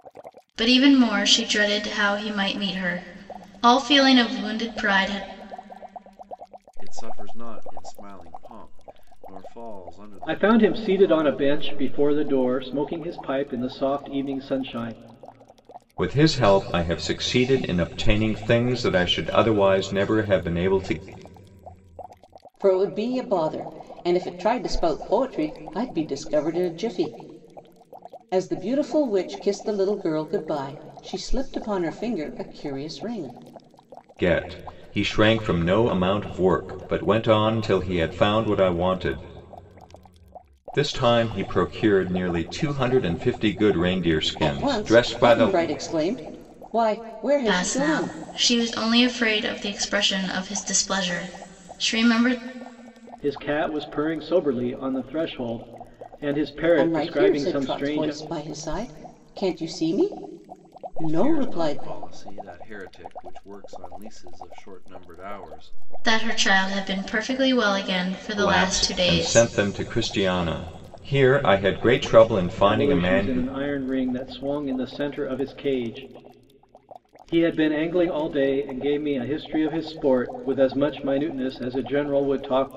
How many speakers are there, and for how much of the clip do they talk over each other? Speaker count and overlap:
5, about 9%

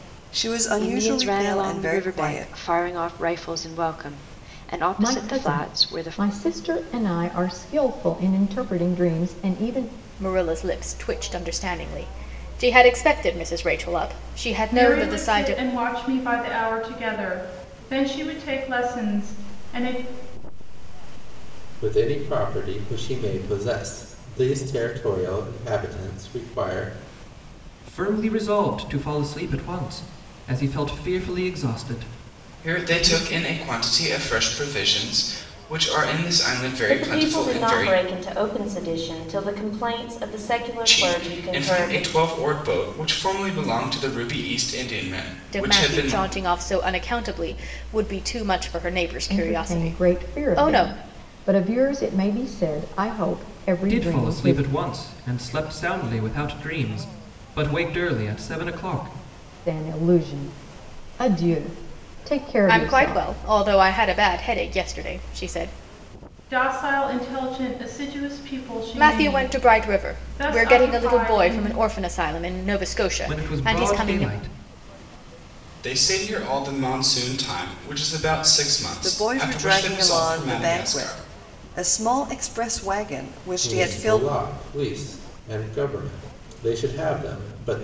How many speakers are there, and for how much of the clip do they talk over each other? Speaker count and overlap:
10, about 23%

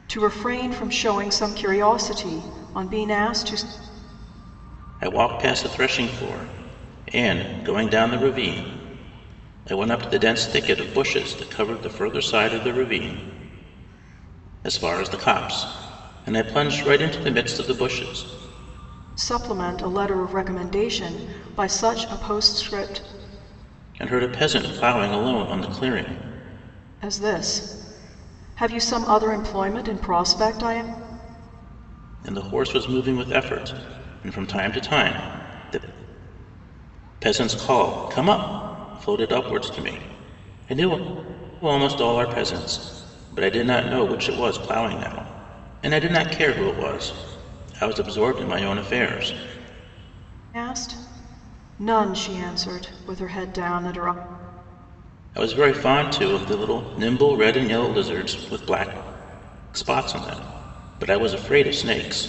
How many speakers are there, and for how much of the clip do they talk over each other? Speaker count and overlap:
2, no overlap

